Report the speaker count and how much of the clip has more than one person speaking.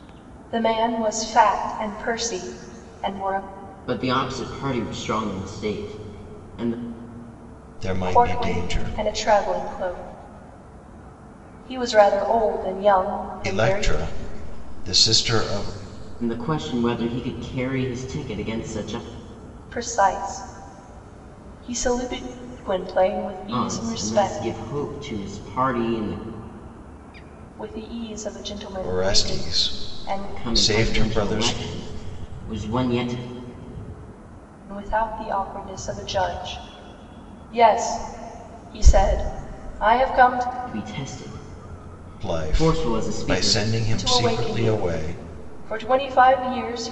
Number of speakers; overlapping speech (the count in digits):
3, about 17%